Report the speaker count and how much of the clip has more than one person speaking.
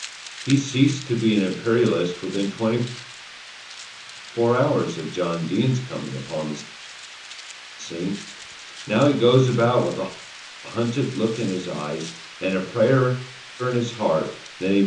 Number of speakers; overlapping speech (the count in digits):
1, no overlap